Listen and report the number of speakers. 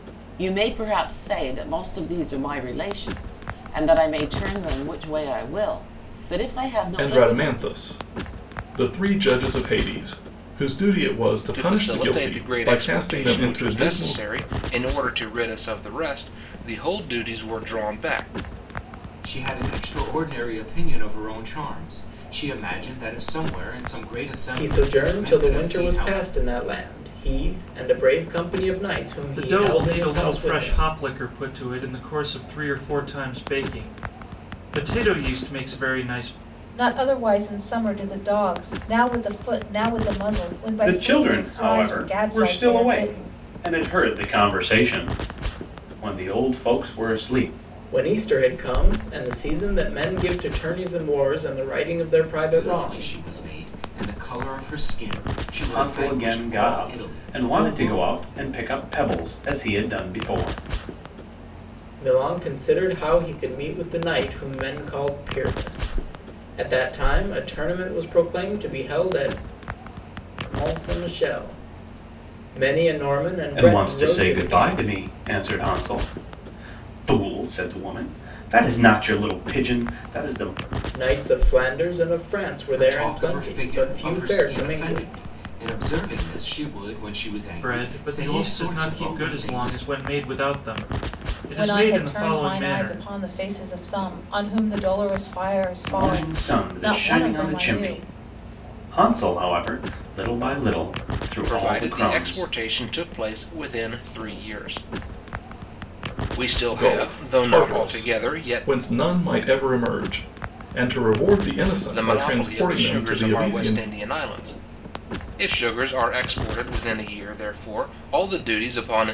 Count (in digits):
8